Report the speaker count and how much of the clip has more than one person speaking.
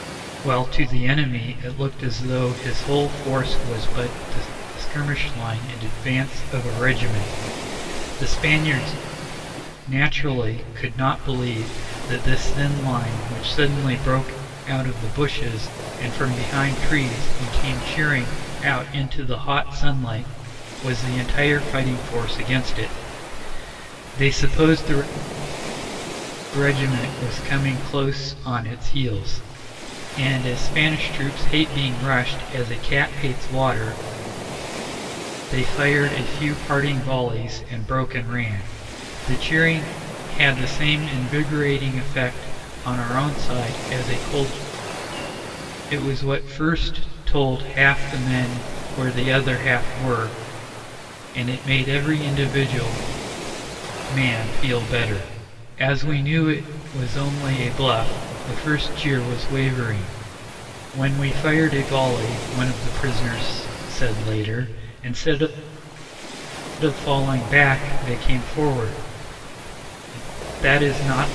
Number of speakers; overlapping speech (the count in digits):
1, no overlap